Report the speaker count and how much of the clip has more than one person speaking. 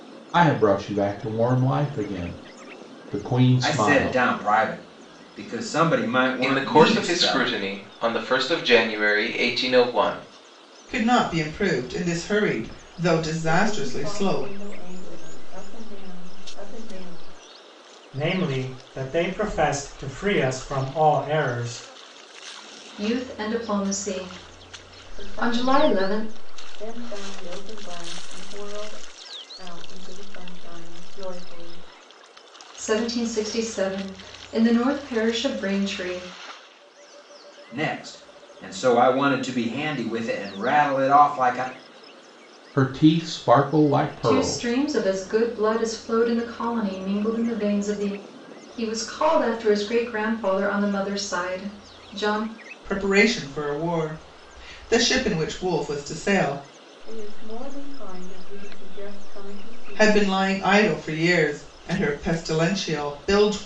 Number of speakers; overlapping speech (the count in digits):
7, about 8%